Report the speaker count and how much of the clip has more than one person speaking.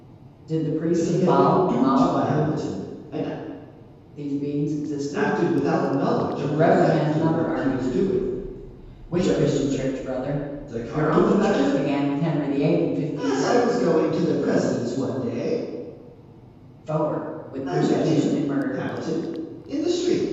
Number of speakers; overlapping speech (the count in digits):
2, about 41%